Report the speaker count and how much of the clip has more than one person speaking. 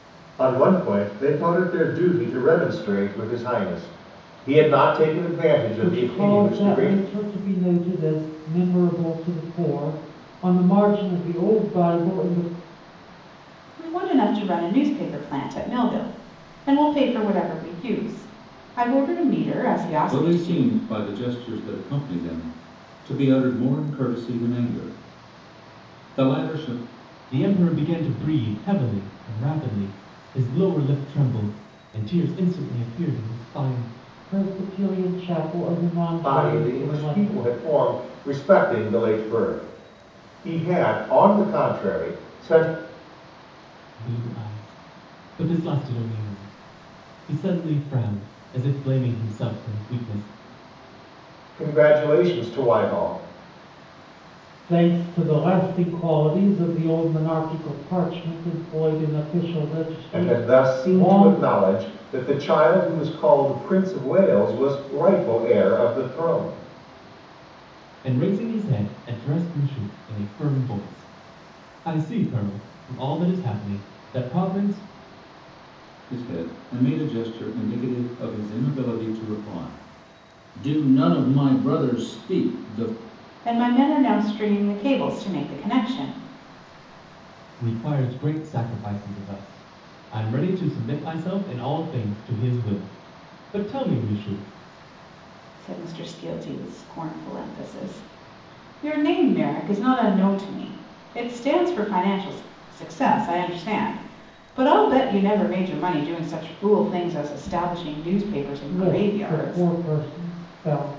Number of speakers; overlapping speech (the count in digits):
5, about 5%